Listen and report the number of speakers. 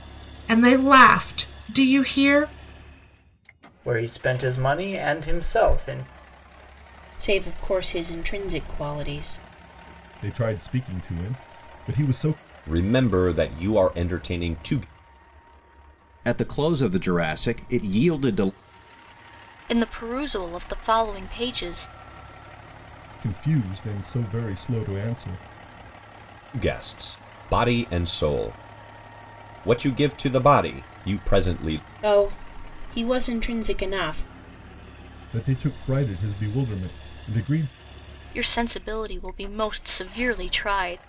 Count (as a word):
seven